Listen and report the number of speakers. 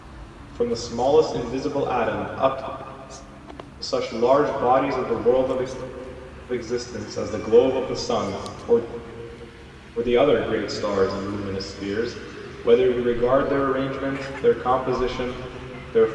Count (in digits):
1